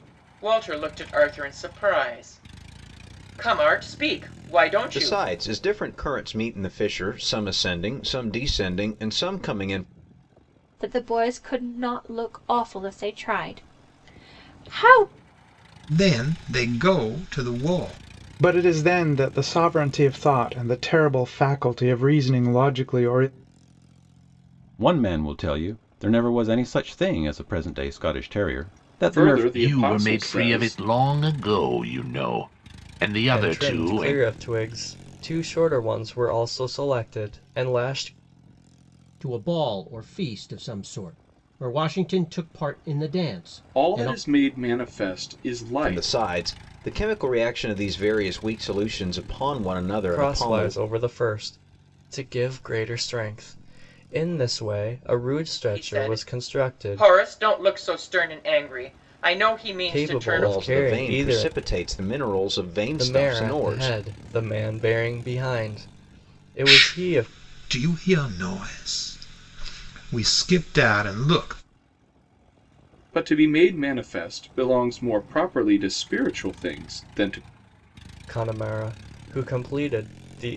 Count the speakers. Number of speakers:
10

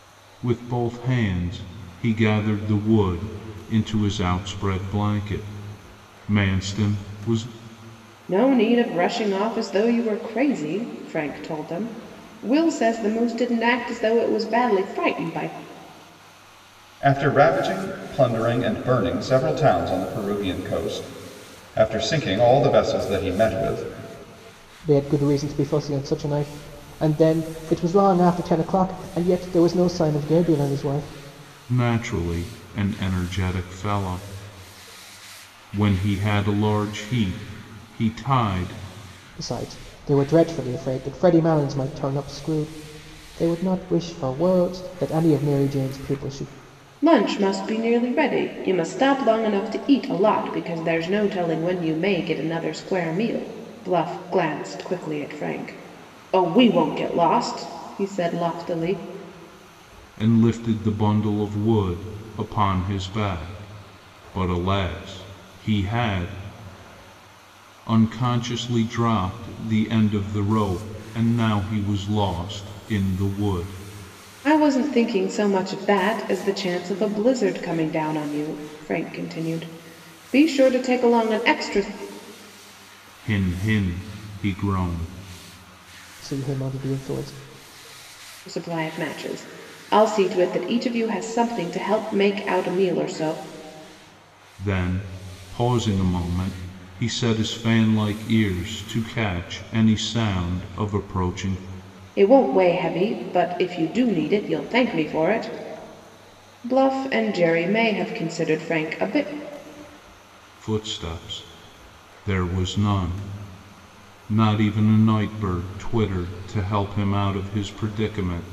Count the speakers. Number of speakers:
4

